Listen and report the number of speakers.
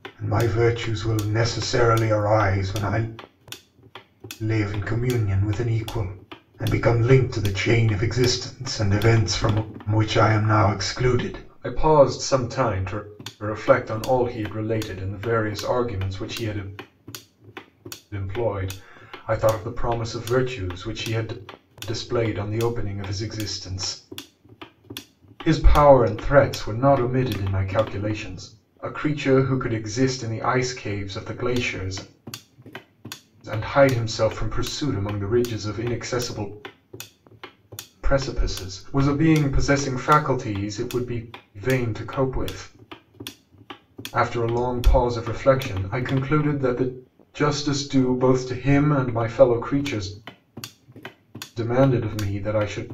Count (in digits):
1